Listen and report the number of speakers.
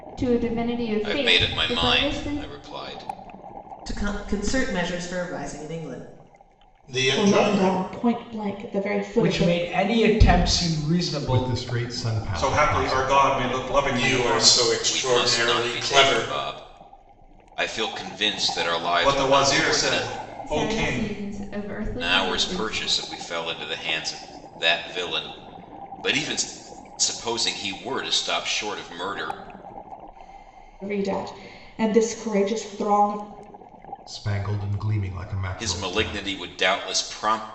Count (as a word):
eight